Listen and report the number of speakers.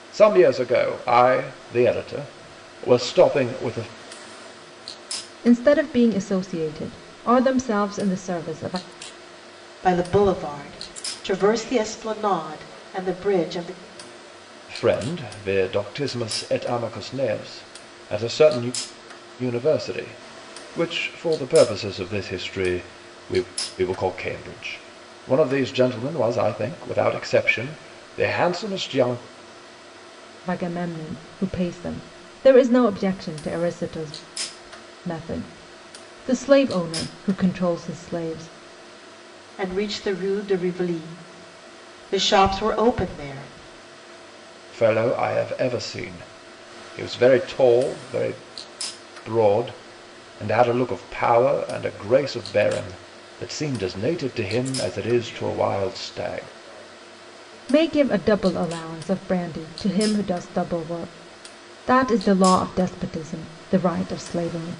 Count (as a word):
three